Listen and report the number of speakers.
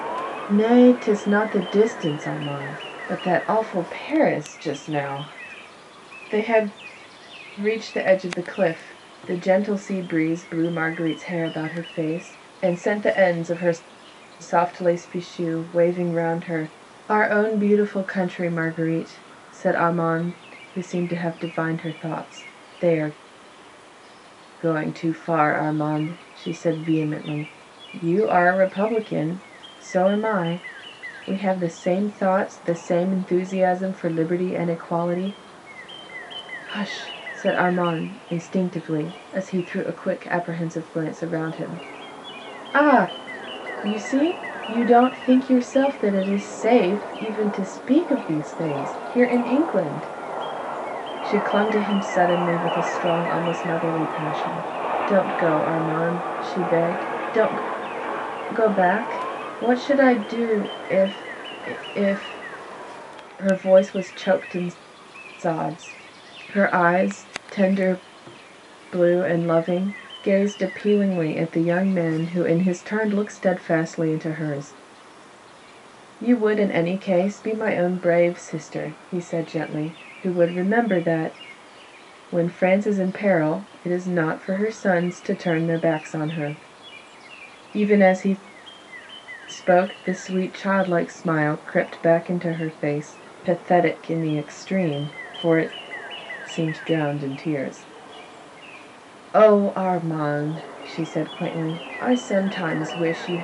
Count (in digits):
1